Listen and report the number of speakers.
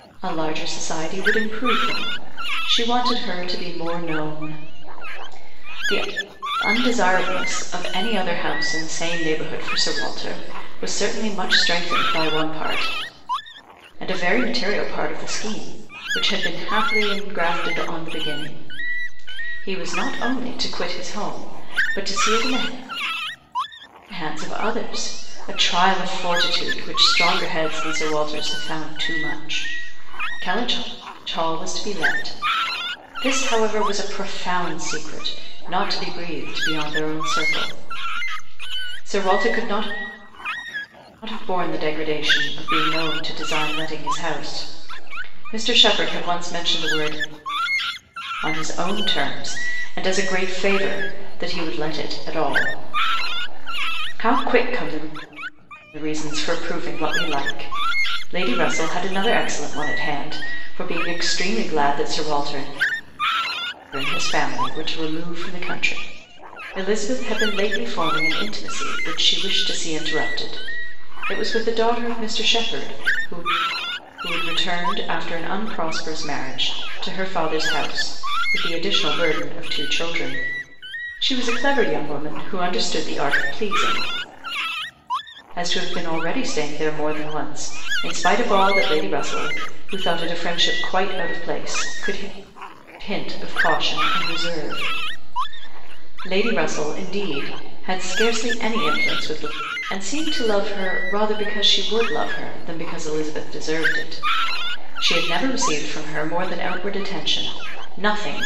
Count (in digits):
1